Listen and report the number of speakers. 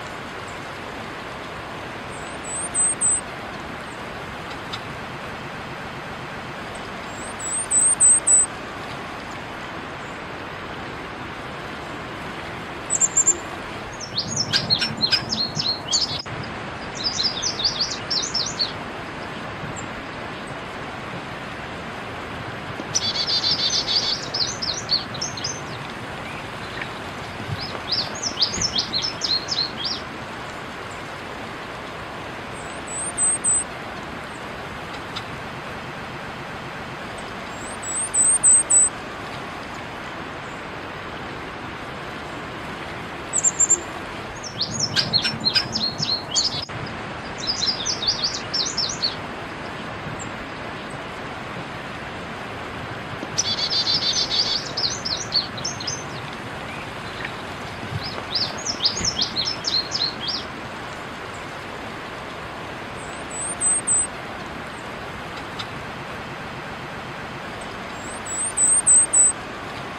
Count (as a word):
zero